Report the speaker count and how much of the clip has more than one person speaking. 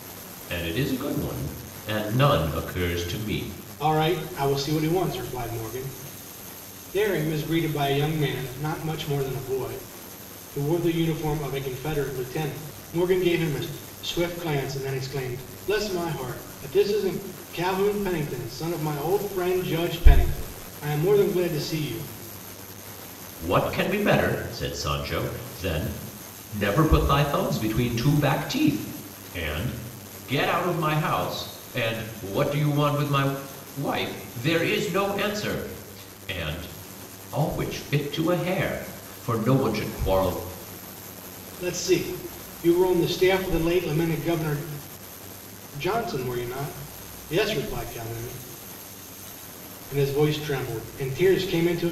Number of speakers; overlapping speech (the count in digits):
2, no overlap